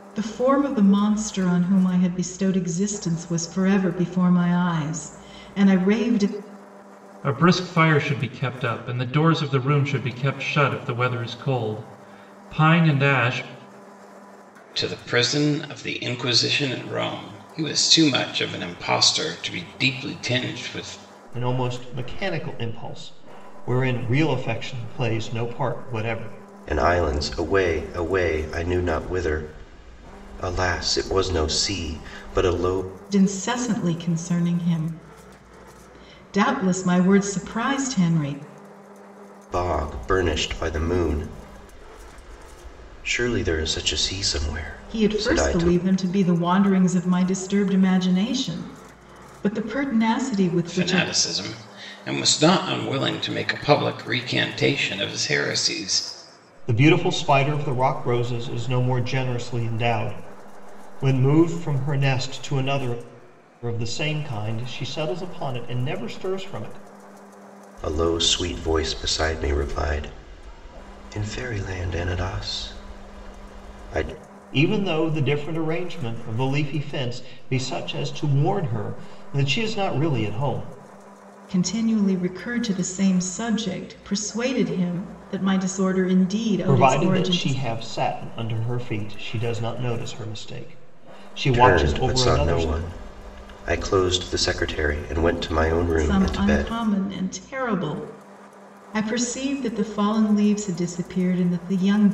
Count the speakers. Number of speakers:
5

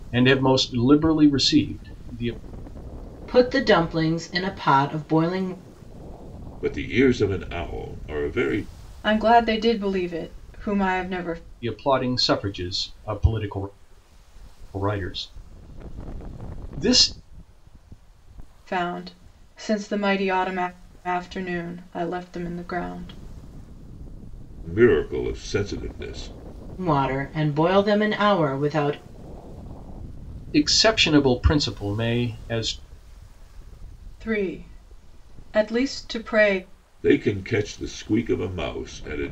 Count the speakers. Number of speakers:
4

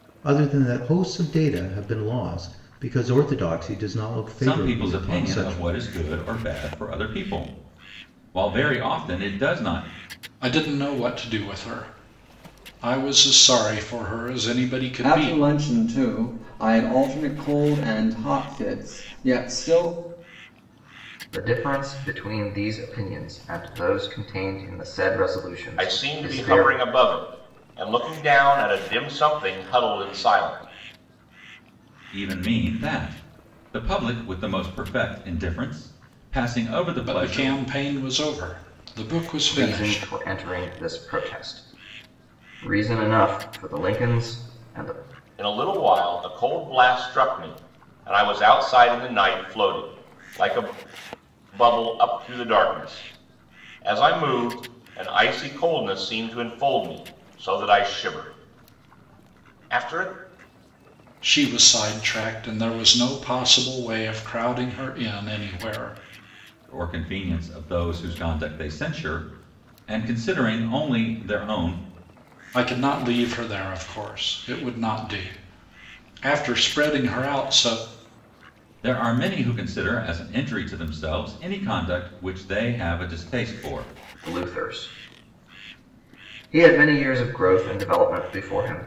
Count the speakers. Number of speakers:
6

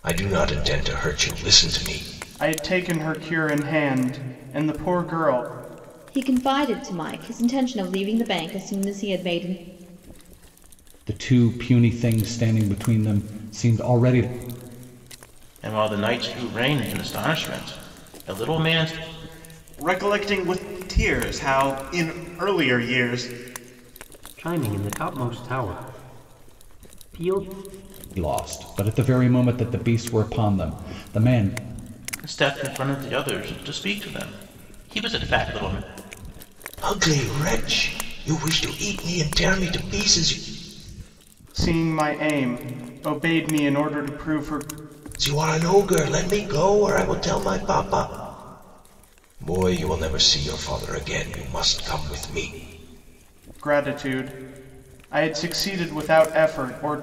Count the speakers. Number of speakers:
7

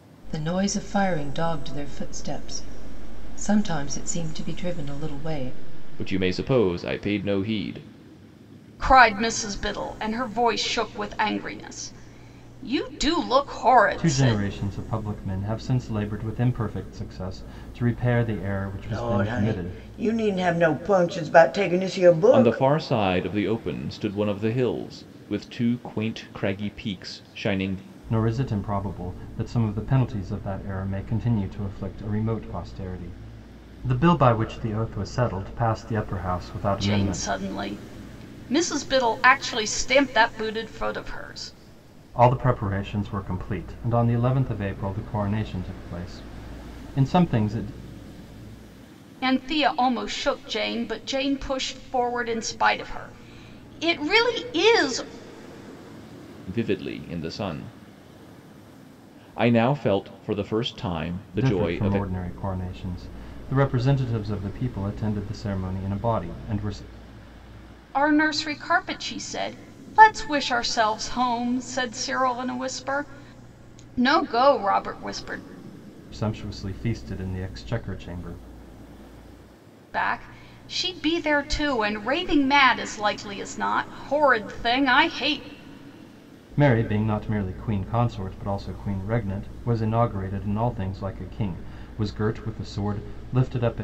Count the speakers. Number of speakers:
5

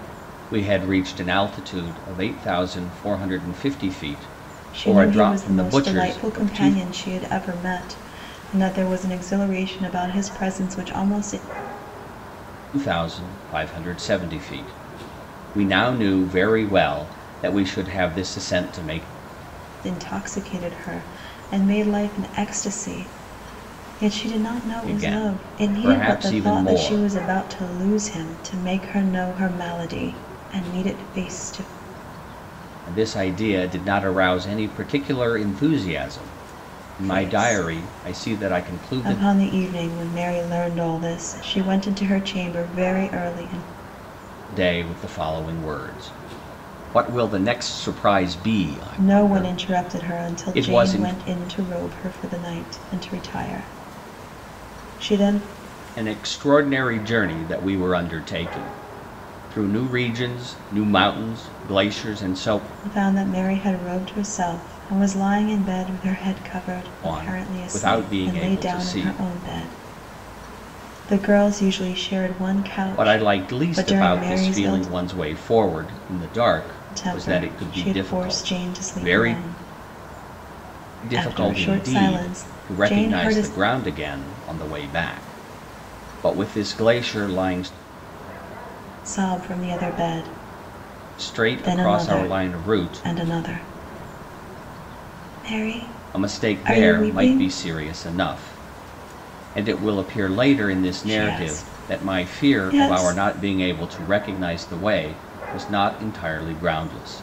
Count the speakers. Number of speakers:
2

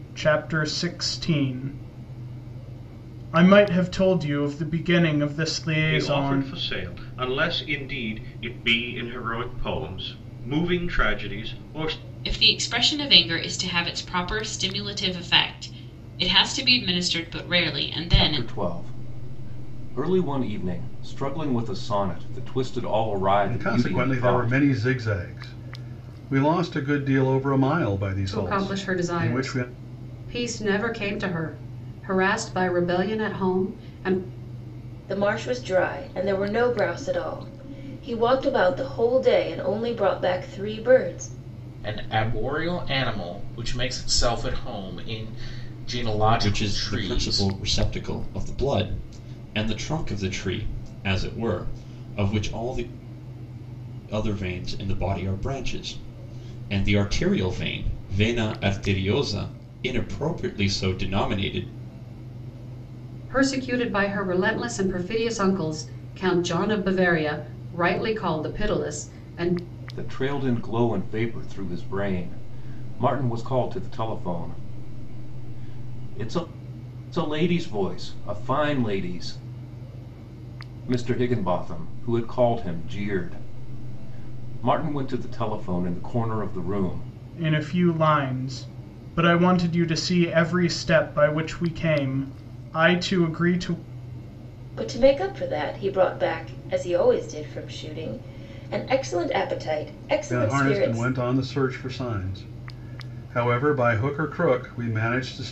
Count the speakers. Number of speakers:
9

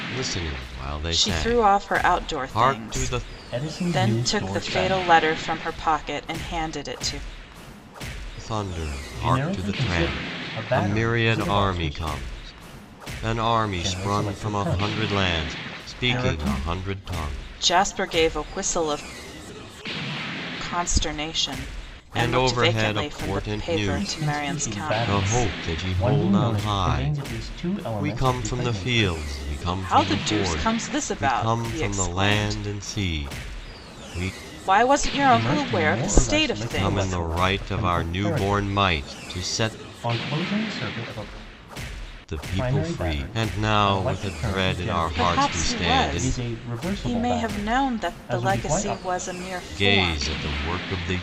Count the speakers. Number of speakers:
3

